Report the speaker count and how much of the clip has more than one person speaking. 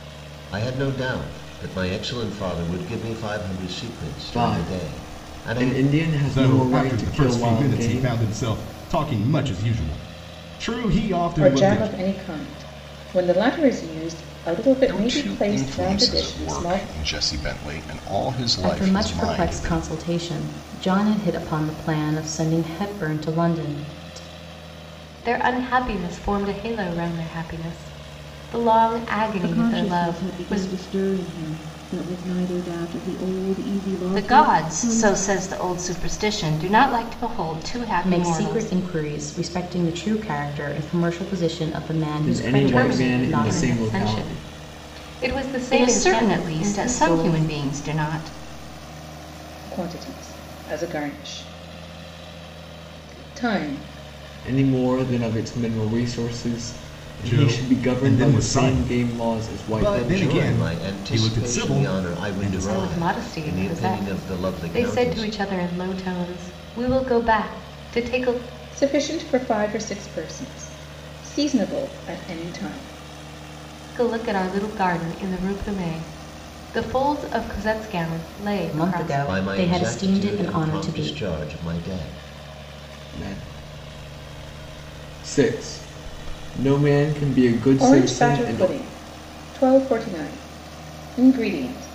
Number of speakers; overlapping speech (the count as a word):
nine, about 28%